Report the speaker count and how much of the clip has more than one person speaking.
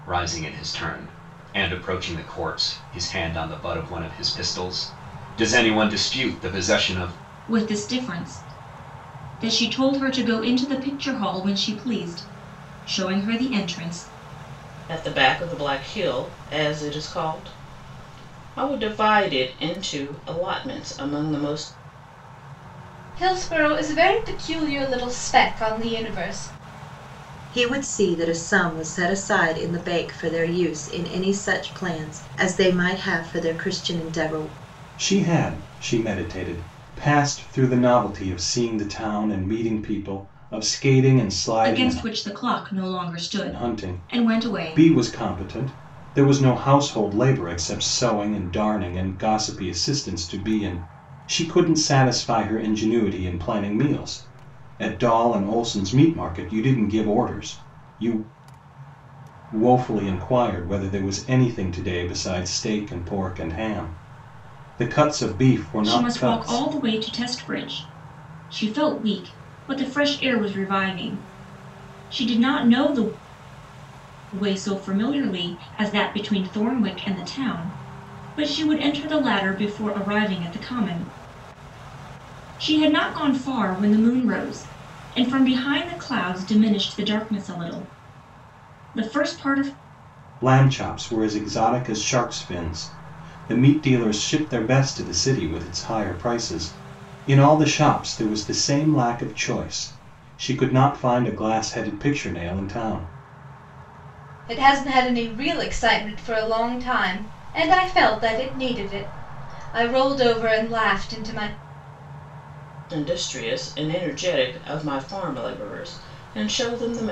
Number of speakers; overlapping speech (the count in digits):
6, about 2%